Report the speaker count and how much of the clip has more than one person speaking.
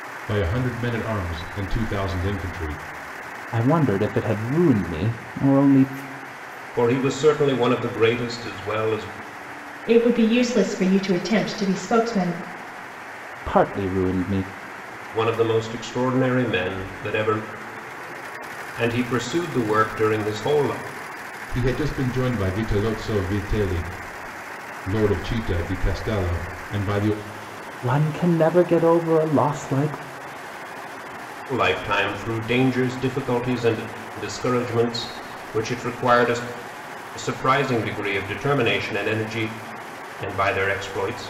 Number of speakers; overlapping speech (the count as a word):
four, no overlap